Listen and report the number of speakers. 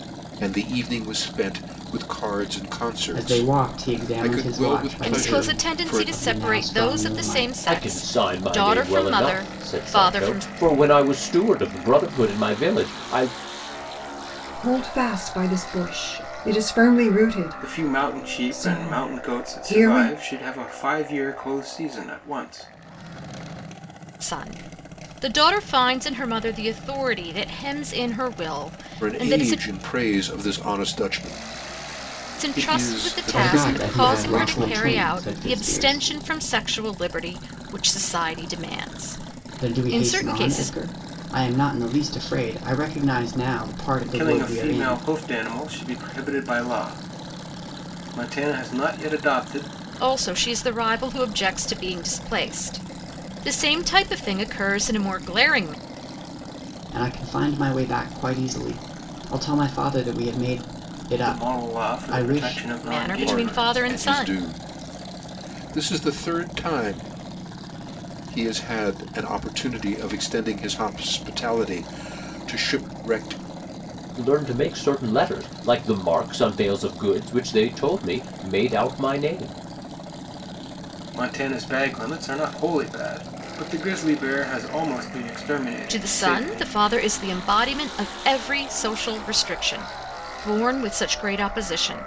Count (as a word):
six